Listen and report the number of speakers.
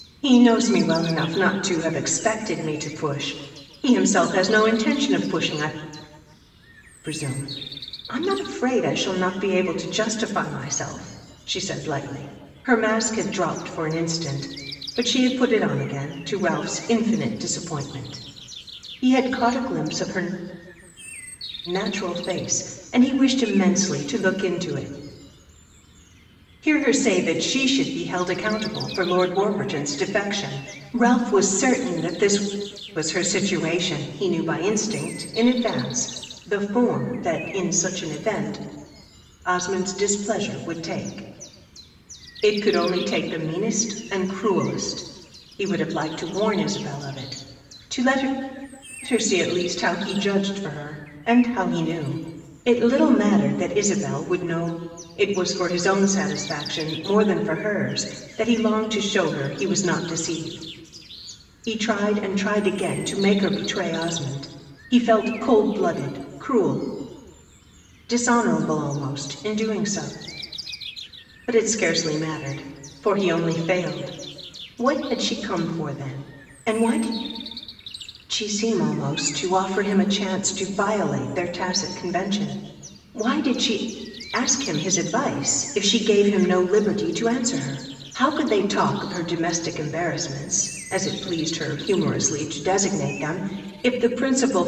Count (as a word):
one